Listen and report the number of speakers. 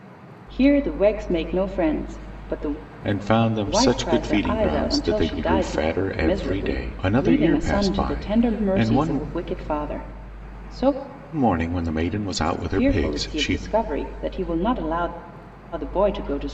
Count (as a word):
two